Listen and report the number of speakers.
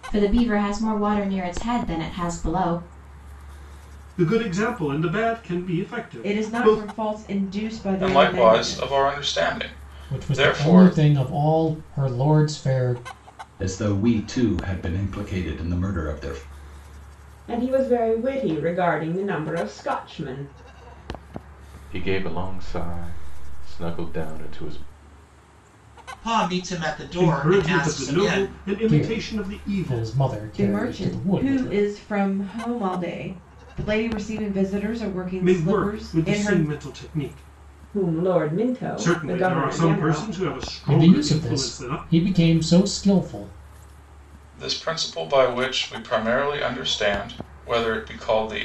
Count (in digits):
9